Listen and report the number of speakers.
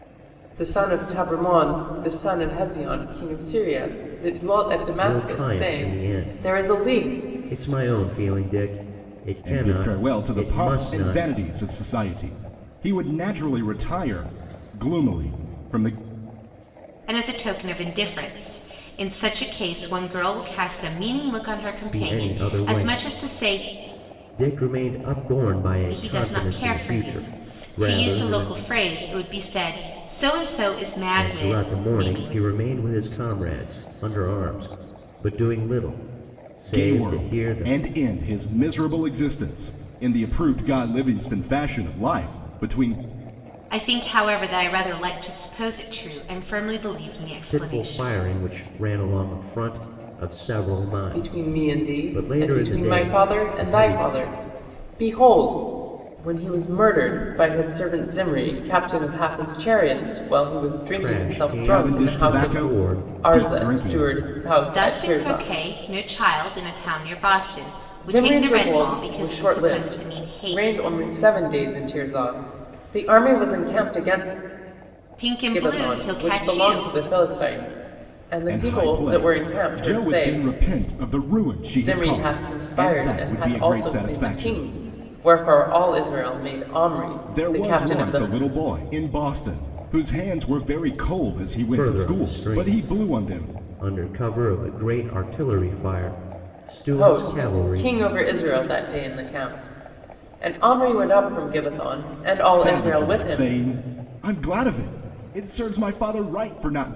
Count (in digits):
4